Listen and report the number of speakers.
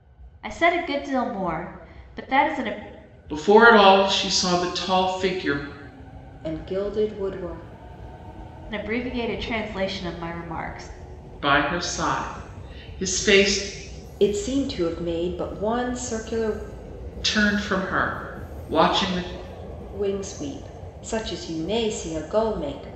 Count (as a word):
three